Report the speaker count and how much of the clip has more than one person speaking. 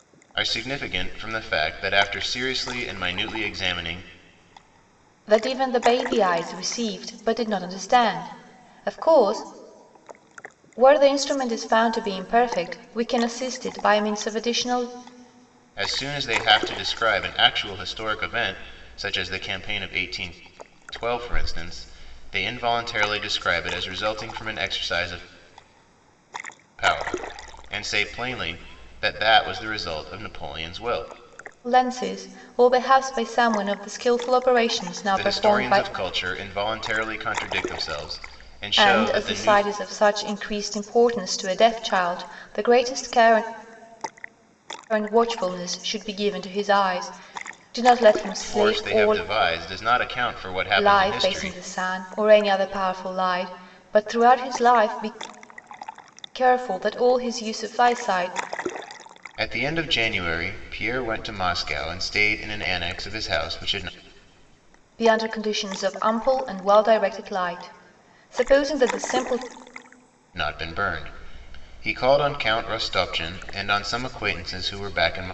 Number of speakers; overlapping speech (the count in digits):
2, about 4%